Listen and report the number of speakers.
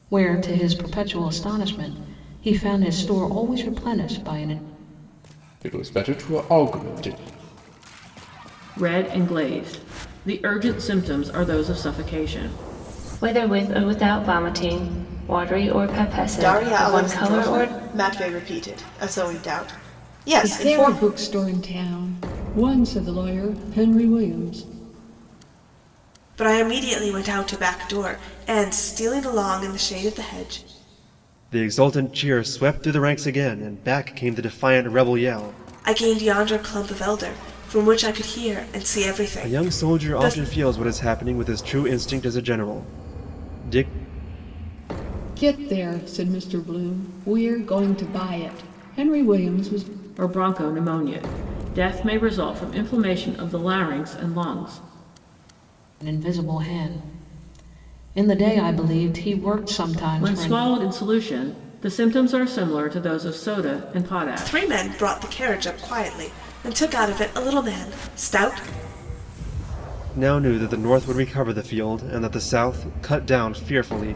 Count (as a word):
eight